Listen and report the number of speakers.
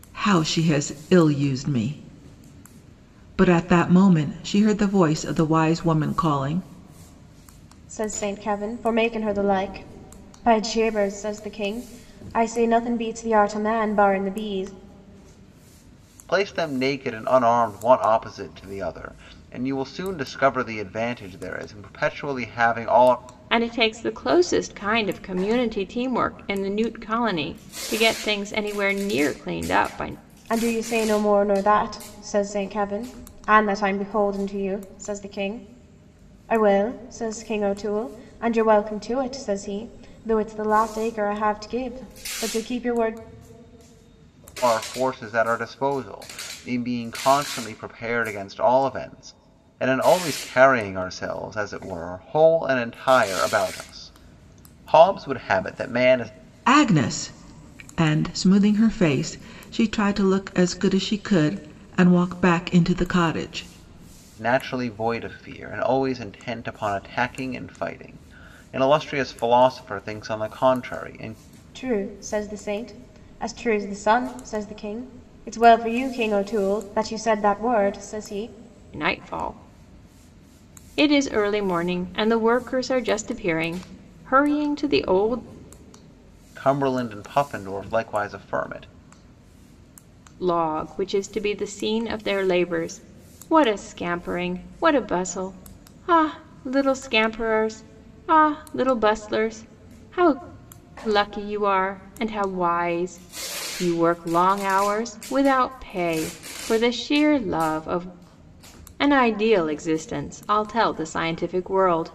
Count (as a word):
four